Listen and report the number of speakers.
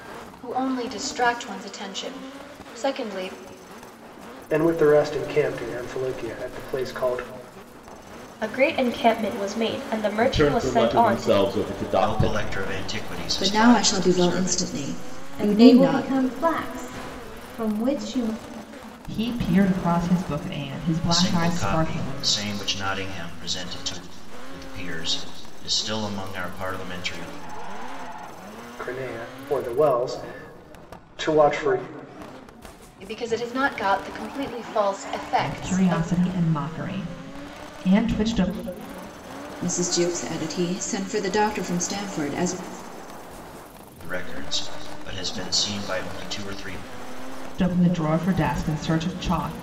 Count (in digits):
8